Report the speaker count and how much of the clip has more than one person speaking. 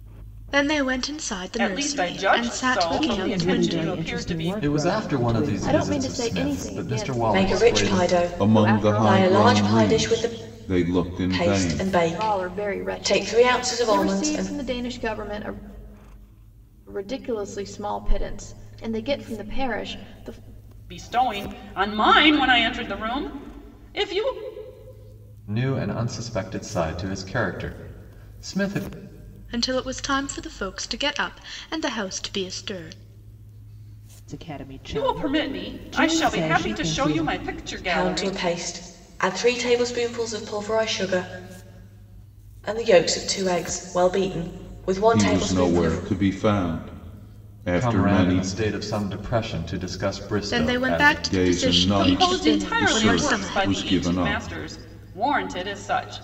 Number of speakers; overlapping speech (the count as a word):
seven, about 36%